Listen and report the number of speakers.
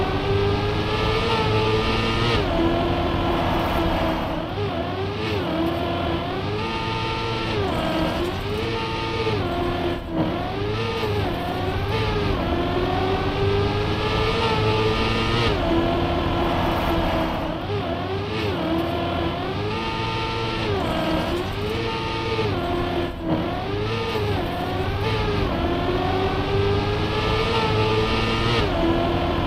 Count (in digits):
0